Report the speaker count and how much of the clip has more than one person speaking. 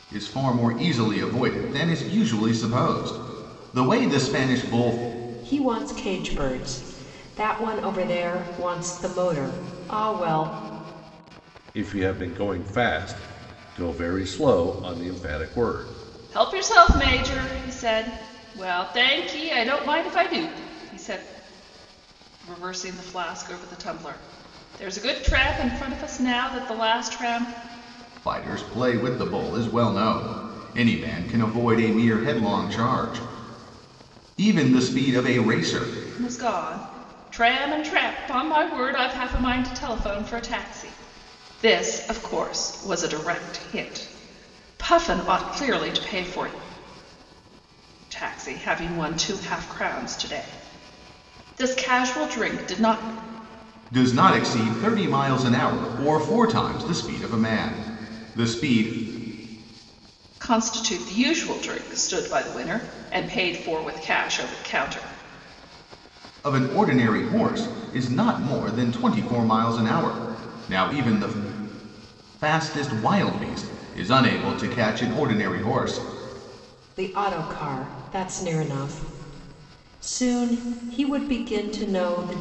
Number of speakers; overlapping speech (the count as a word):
four, no overlap